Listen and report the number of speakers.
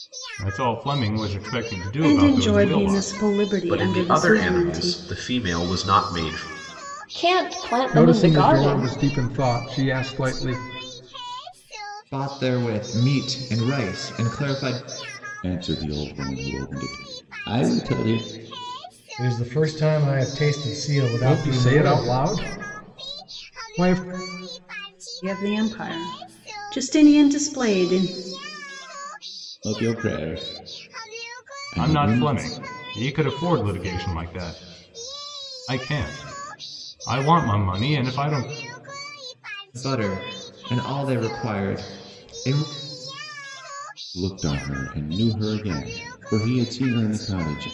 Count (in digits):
8